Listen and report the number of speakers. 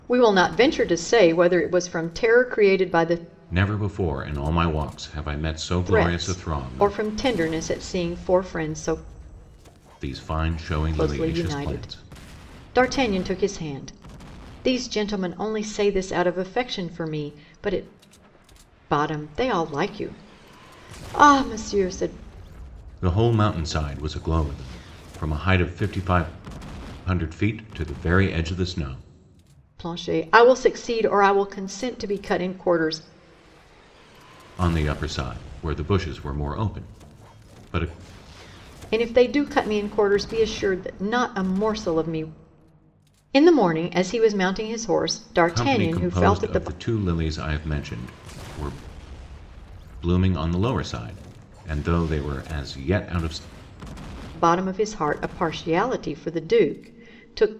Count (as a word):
two